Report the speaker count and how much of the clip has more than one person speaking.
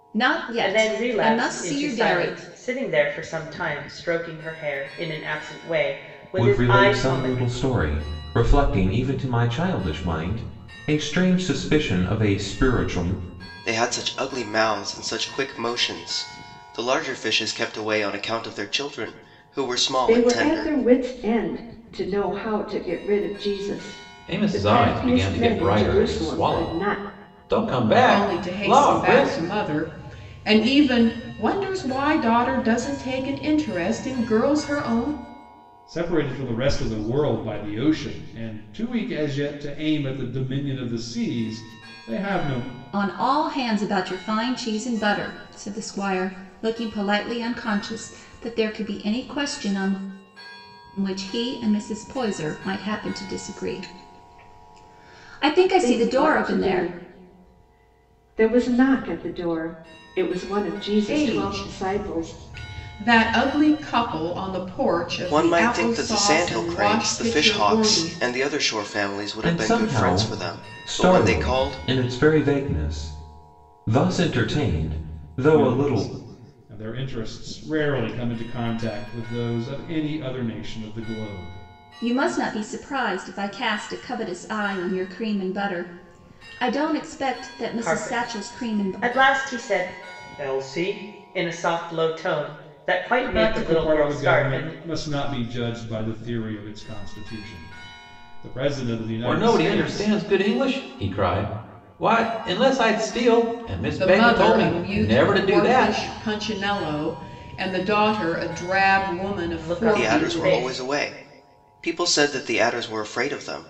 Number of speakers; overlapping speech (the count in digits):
8, about 21%